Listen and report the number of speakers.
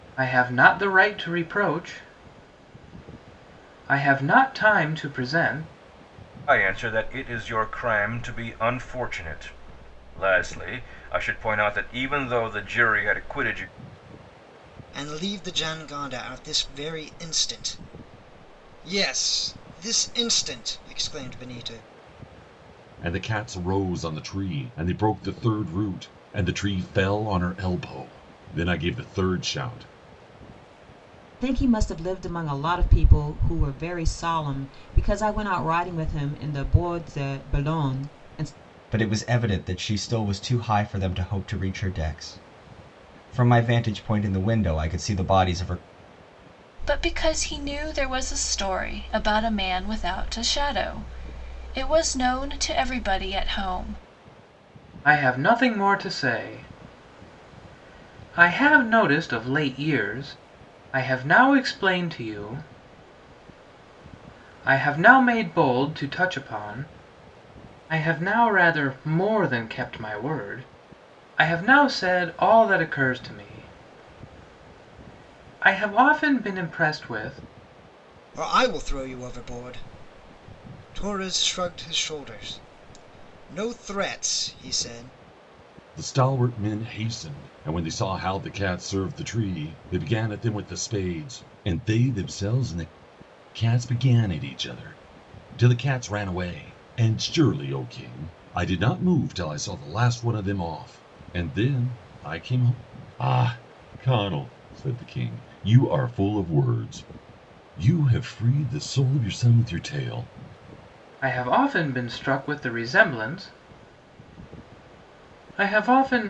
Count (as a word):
seven